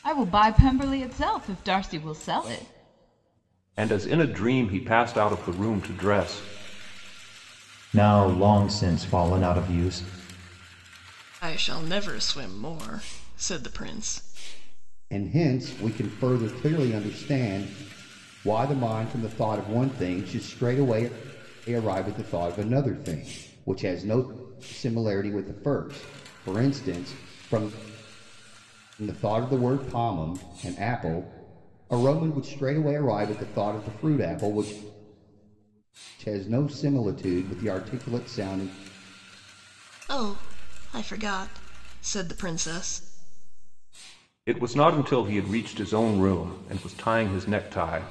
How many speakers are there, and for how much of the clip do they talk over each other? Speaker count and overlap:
5, no overlap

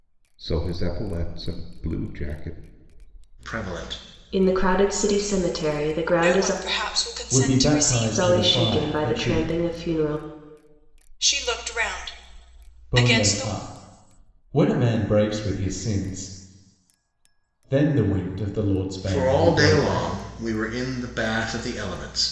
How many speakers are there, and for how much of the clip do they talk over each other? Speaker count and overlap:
5, about 20%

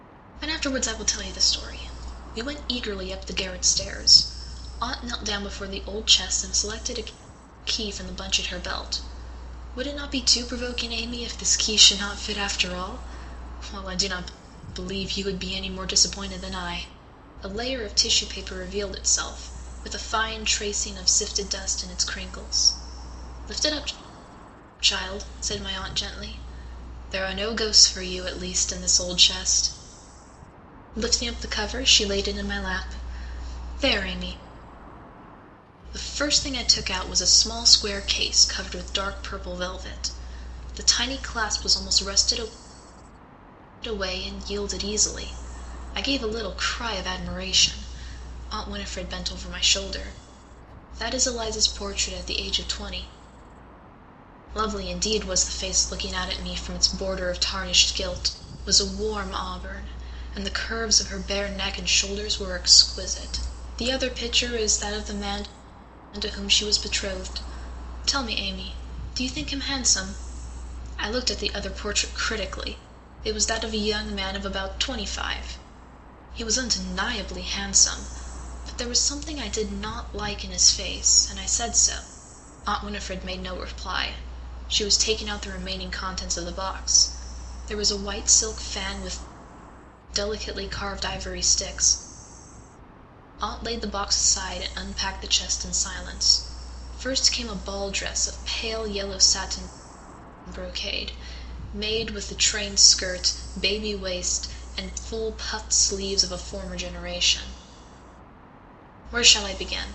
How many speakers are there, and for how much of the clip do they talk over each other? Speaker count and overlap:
1, no overlap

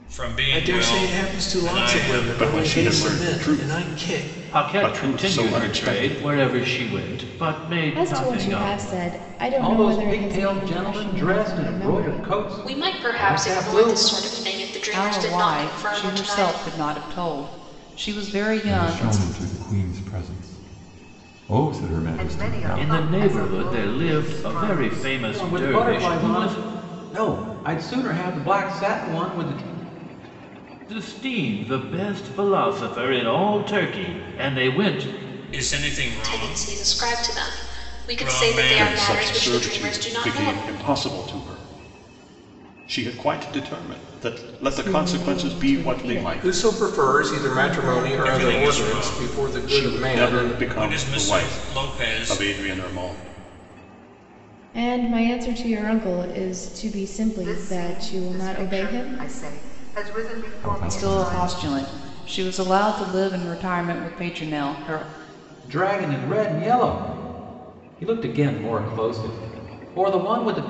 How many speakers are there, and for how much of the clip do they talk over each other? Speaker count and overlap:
10, about 46%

